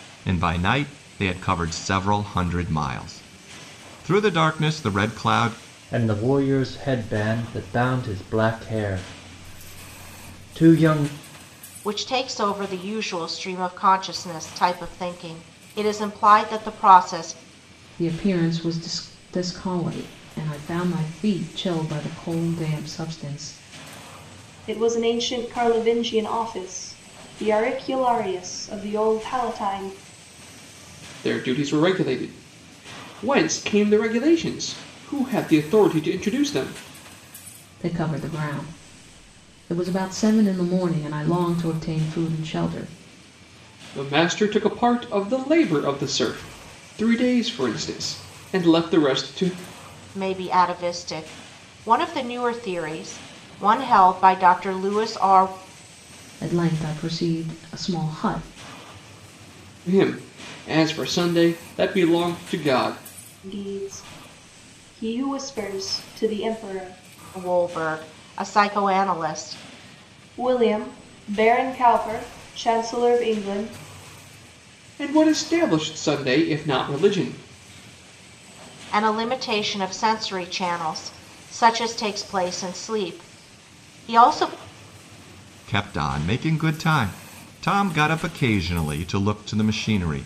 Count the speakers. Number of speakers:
6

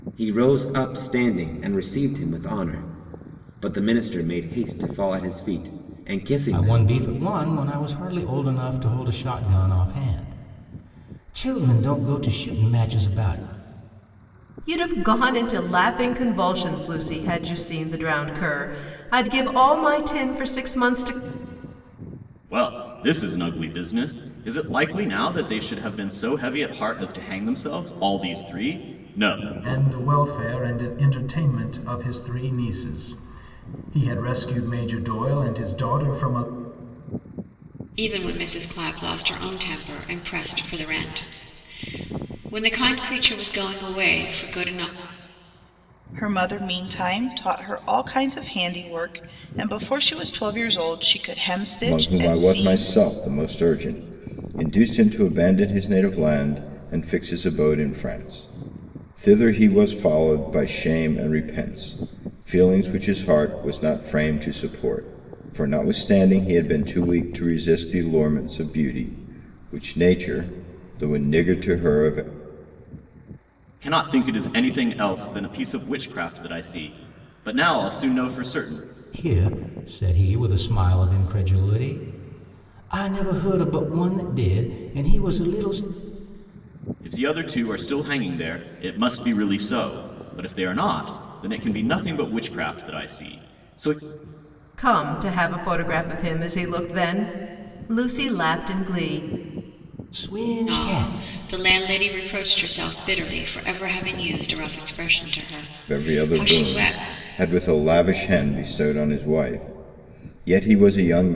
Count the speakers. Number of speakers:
8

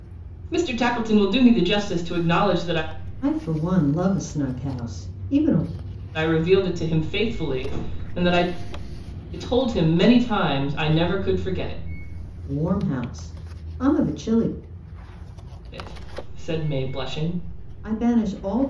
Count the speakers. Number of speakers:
2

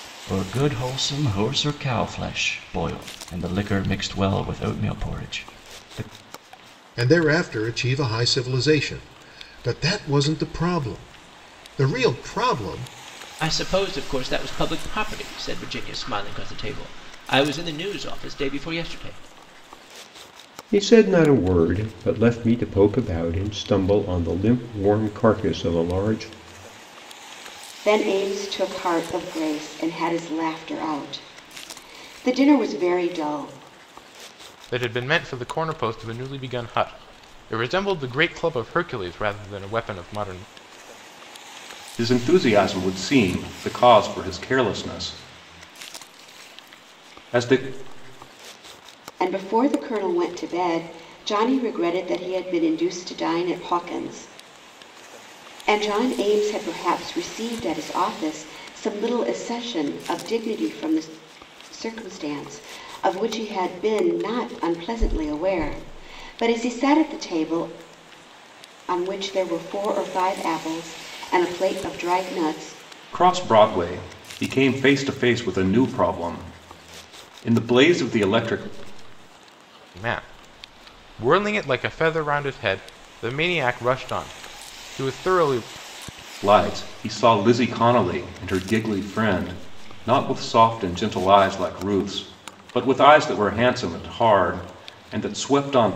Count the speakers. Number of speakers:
7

